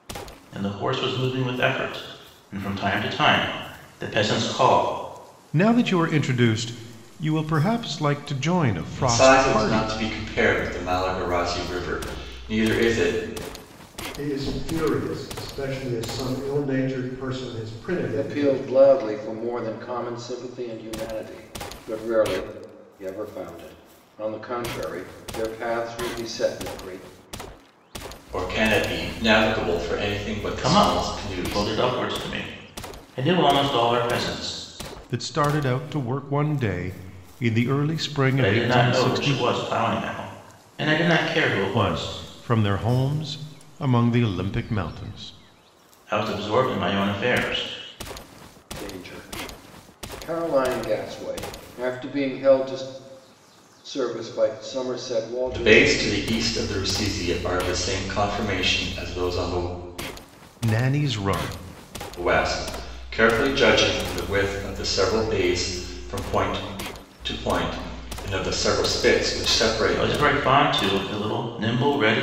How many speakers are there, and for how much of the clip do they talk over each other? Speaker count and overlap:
5, about 7%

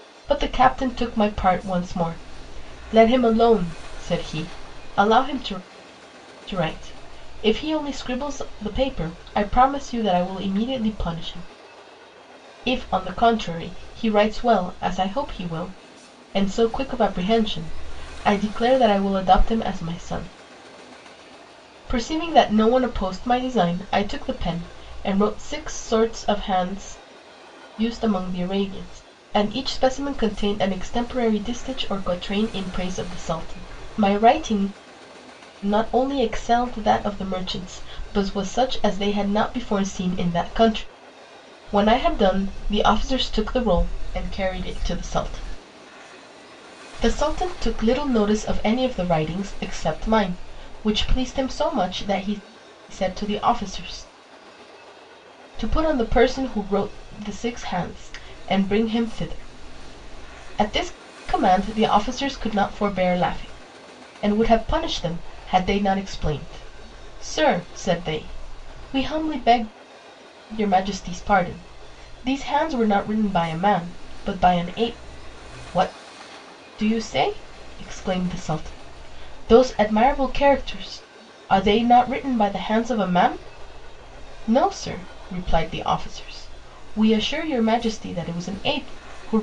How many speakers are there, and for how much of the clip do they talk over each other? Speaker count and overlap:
1, no overlap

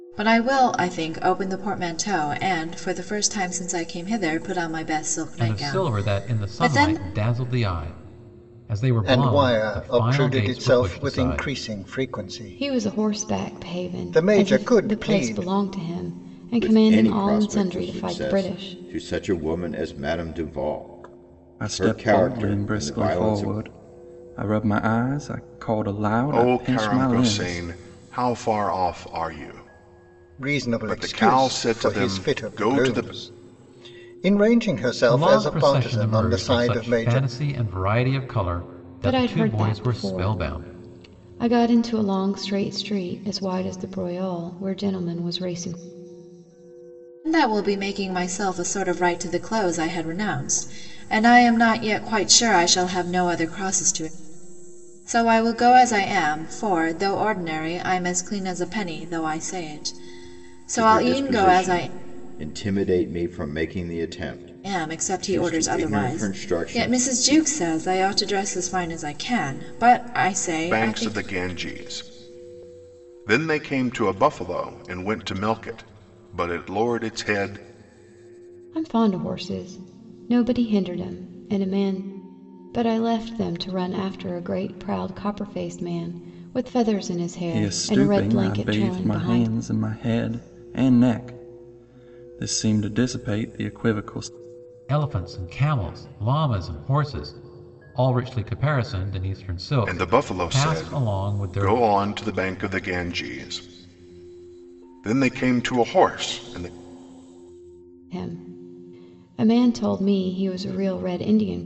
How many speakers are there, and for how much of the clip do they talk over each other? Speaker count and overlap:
7, about 25%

